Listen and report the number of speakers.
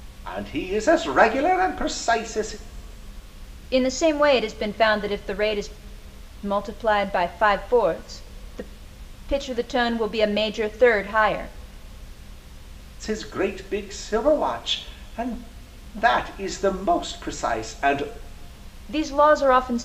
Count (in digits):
2